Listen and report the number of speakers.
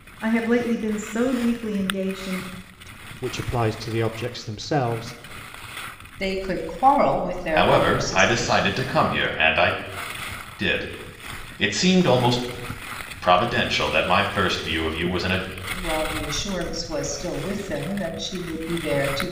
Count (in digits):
4